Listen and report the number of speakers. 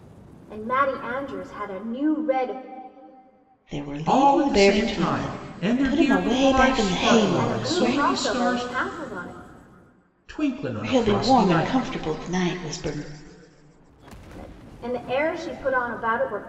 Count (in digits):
3